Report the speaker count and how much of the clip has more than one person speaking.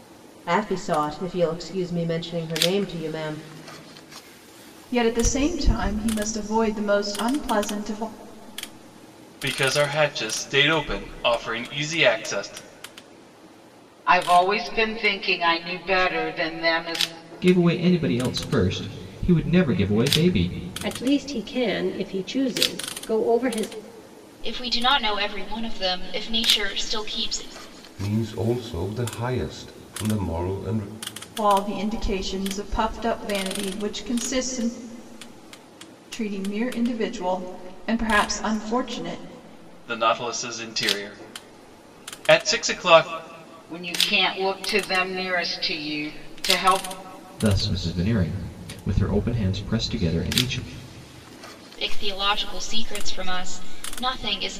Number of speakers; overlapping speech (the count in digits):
8, no overlap